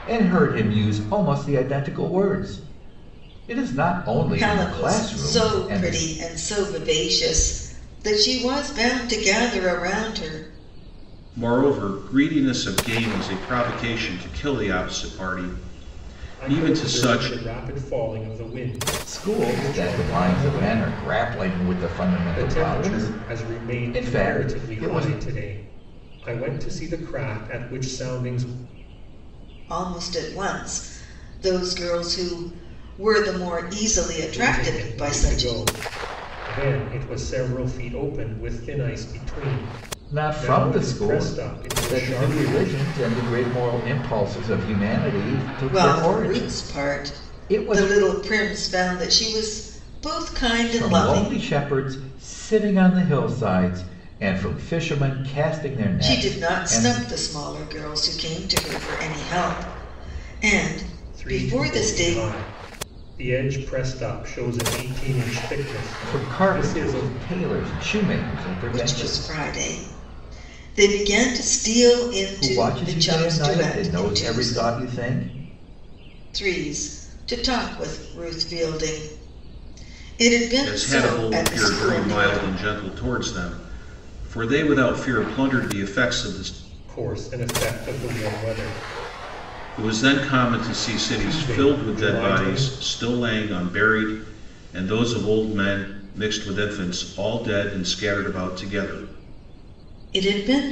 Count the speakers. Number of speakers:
4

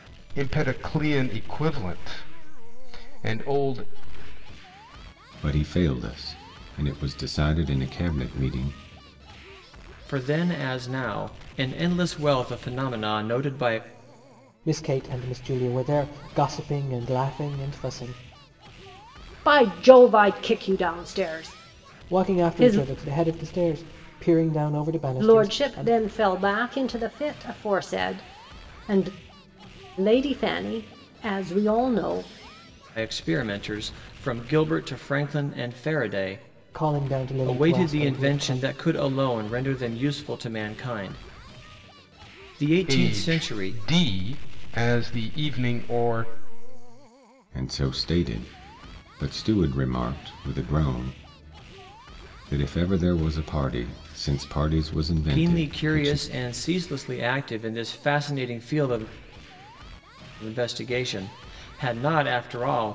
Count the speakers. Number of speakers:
5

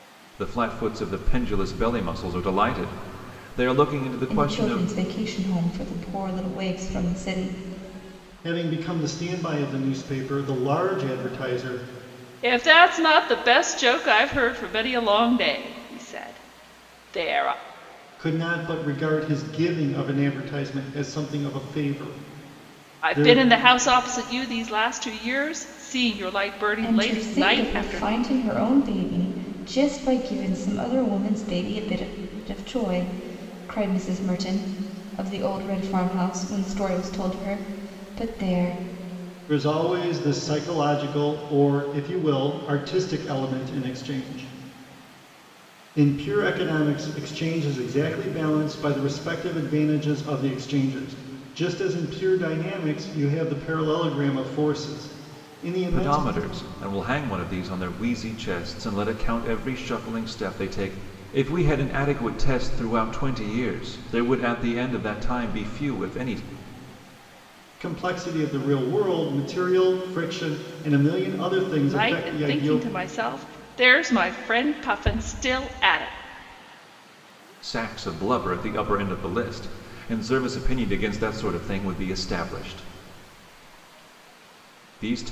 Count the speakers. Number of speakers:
4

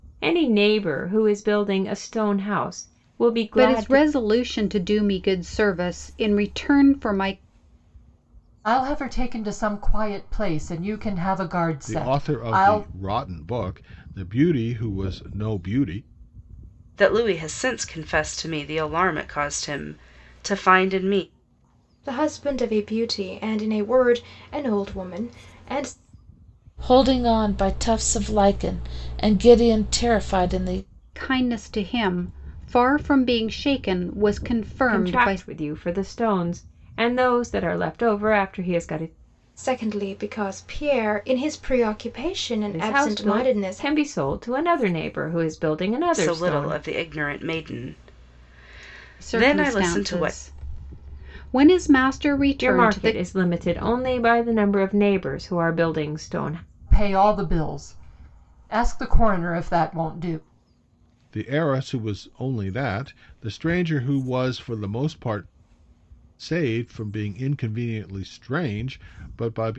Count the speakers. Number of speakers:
7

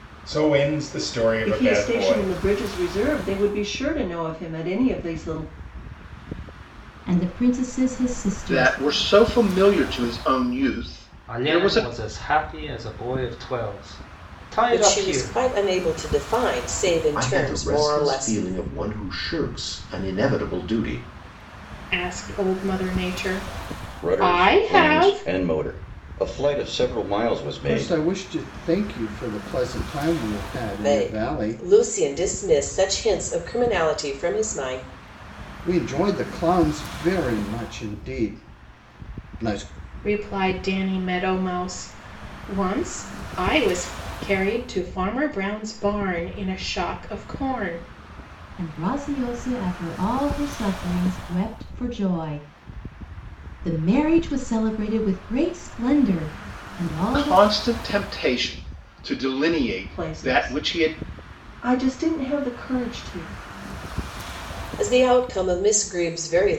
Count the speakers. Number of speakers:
10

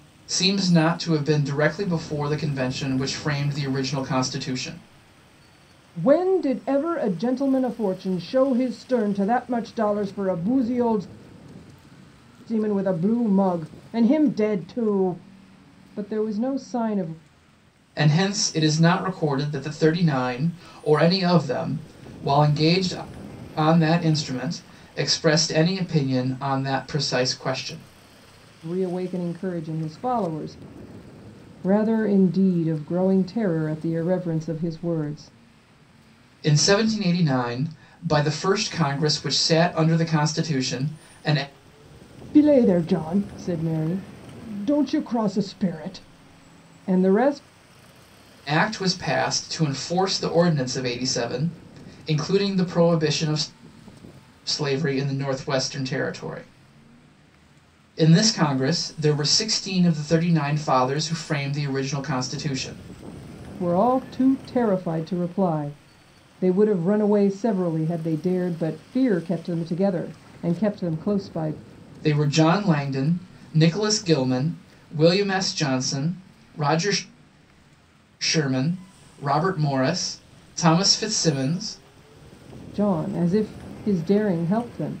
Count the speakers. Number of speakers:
2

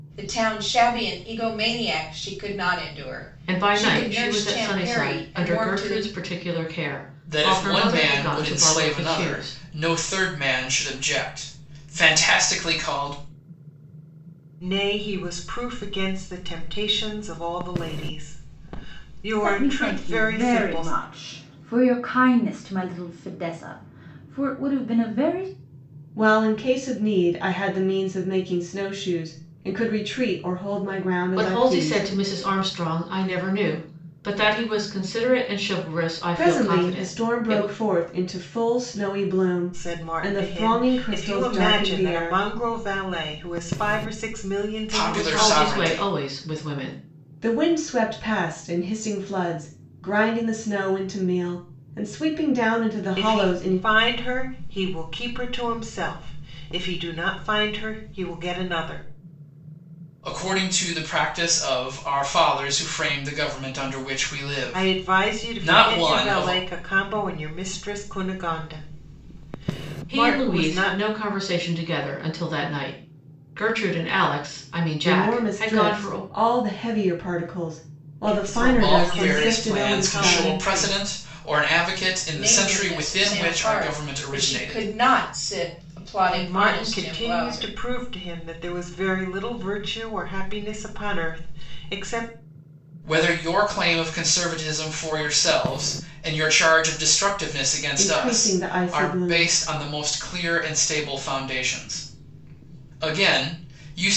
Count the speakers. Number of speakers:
6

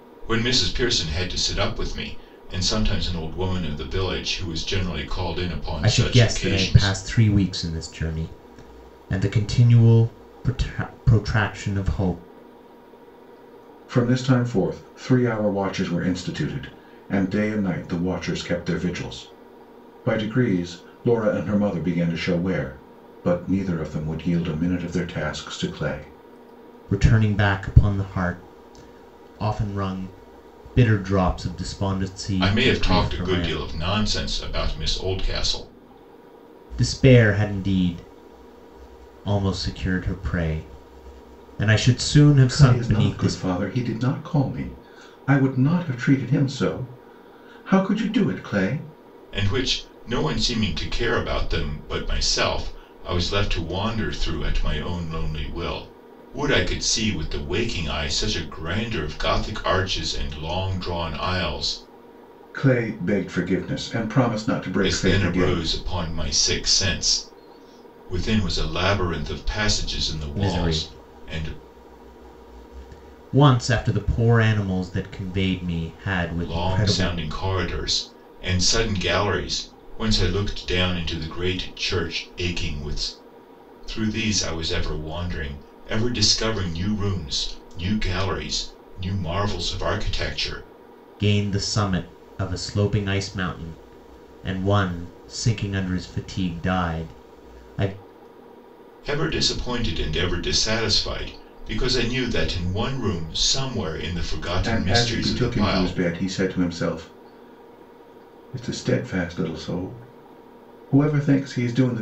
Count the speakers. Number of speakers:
3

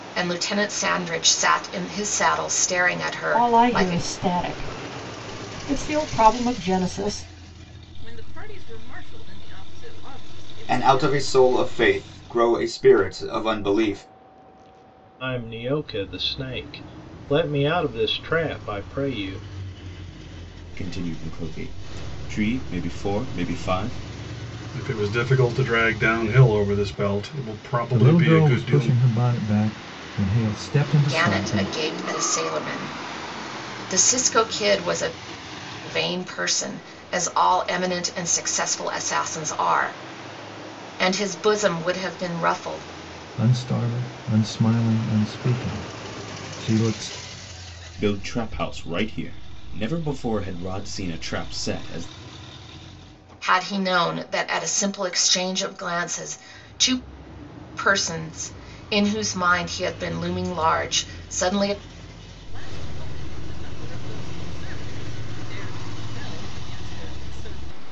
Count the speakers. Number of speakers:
8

